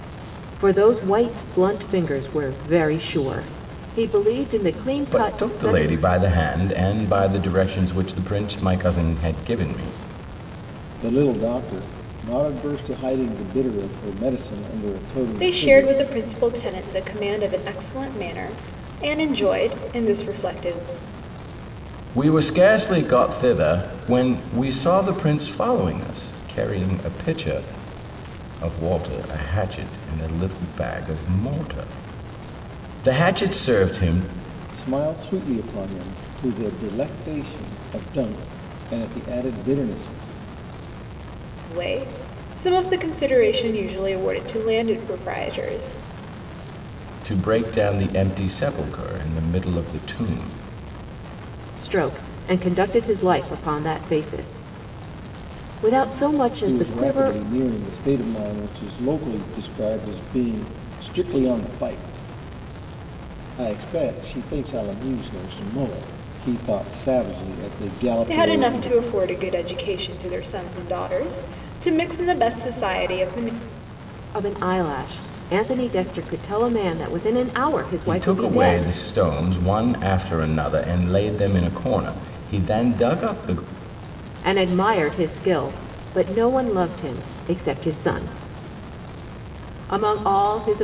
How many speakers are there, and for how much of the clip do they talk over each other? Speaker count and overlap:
4, about 5%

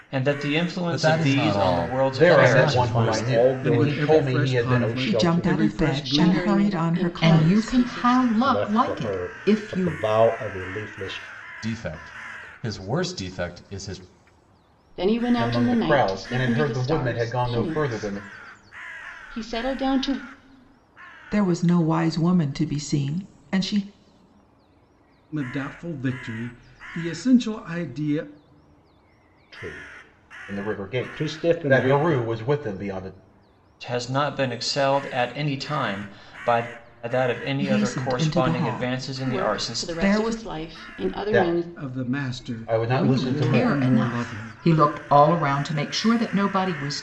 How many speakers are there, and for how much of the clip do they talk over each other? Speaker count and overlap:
8, about 42%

